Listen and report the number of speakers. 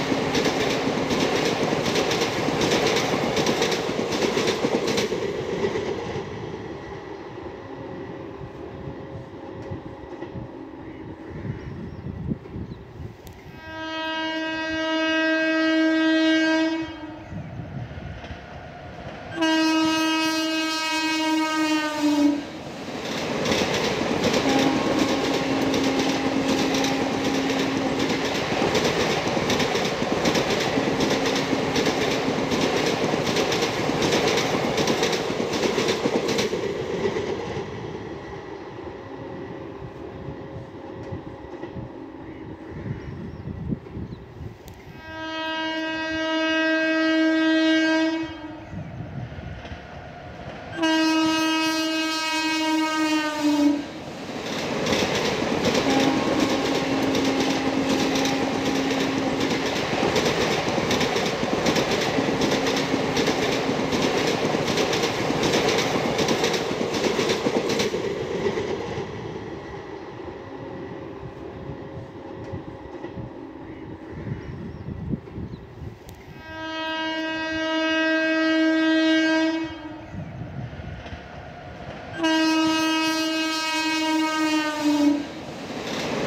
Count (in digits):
0